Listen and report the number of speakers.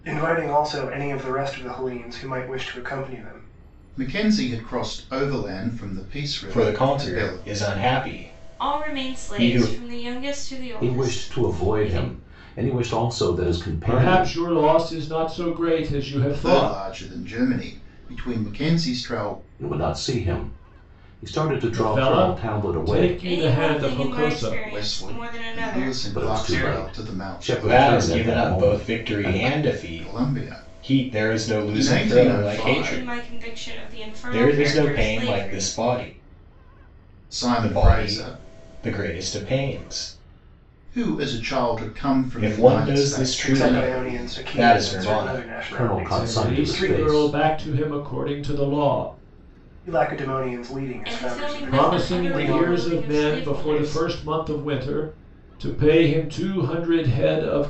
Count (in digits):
6